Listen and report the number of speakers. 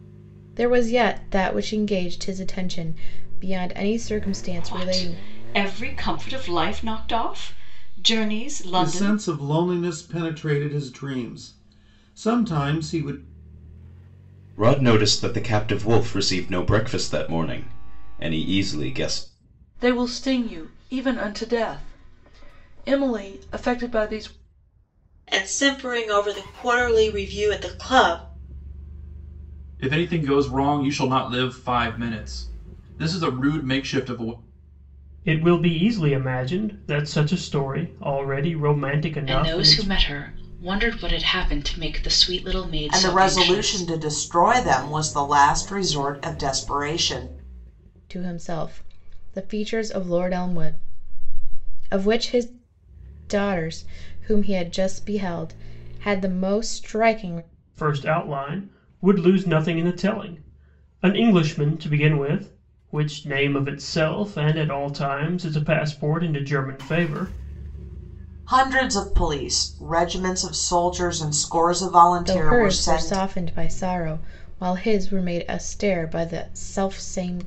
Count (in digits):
10